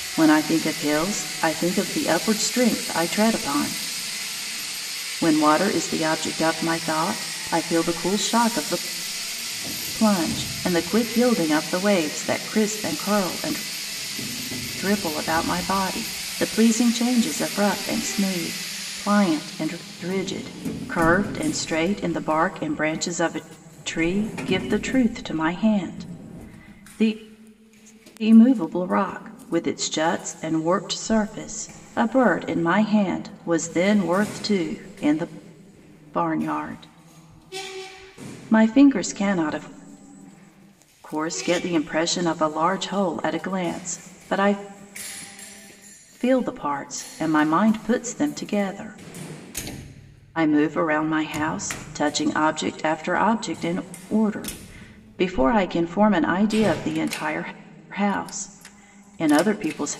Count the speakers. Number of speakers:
one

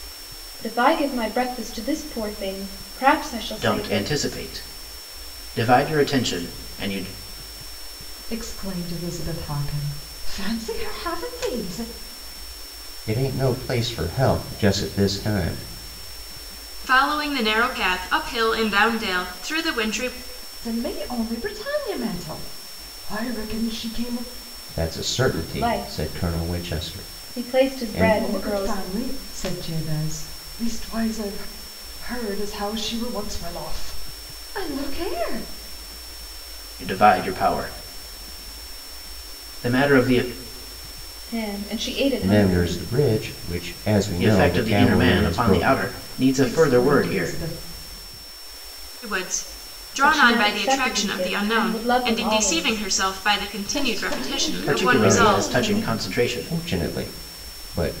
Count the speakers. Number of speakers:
five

